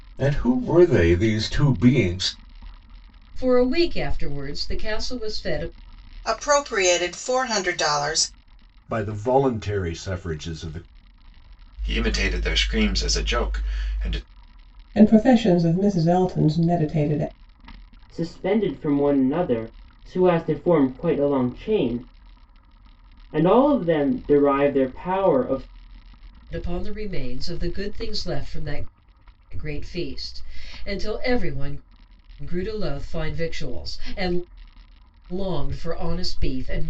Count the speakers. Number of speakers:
seven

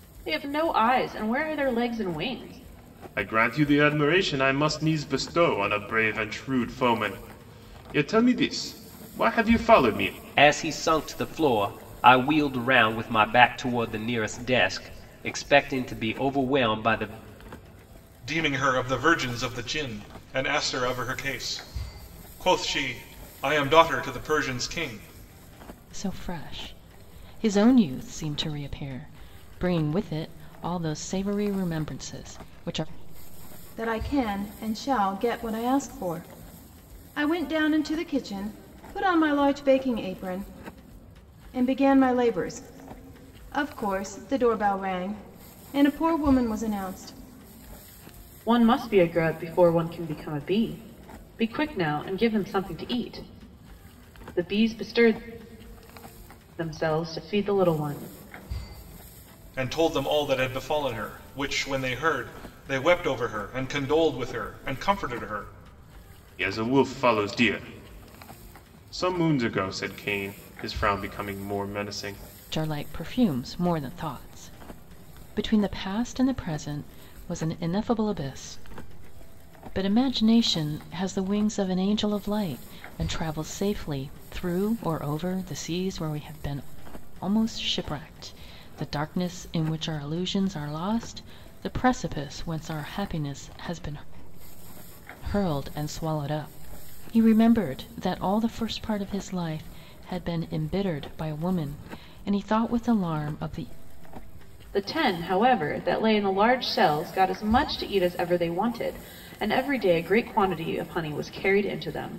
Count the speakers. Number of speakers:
six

